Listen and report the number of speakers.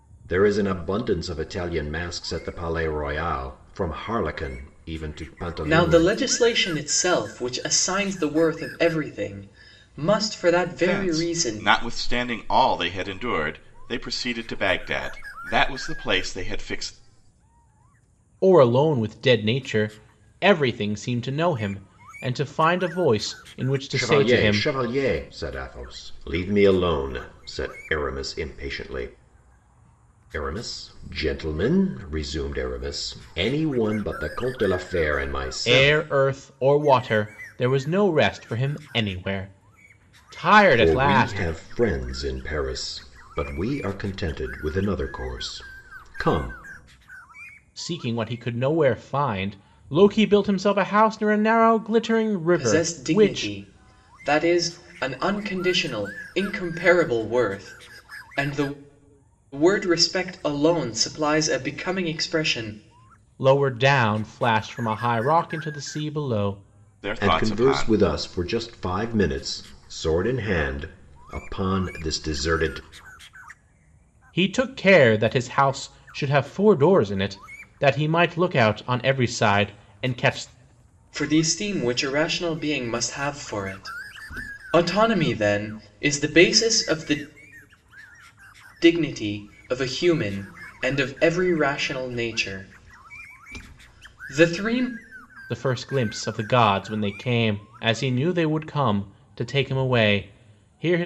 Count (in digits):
4